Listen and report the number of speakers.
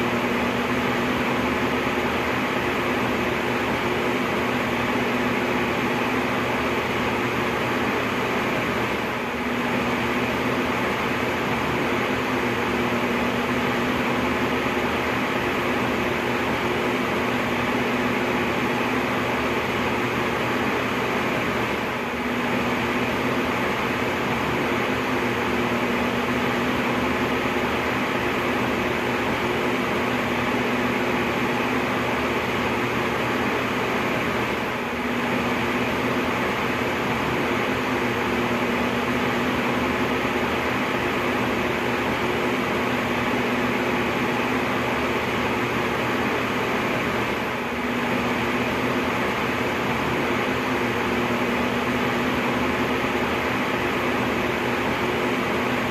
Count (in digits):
0